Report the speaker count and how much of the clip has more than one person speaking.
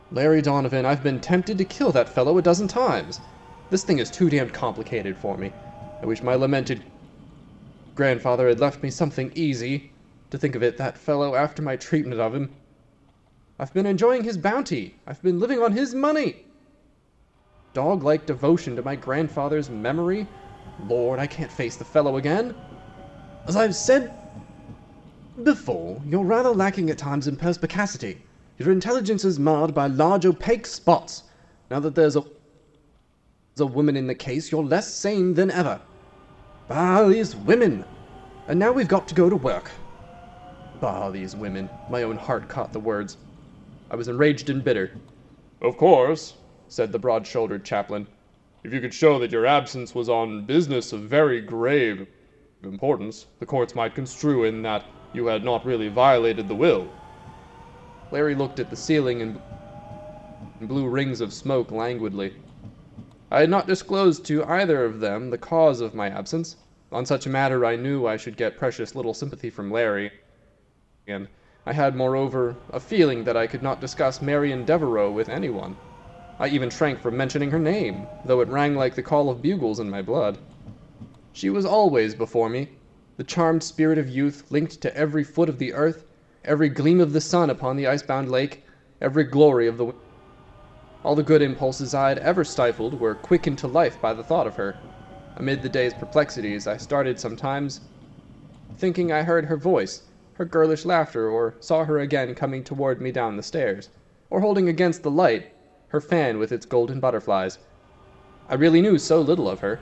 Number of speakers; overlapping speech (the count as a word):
one, no overlap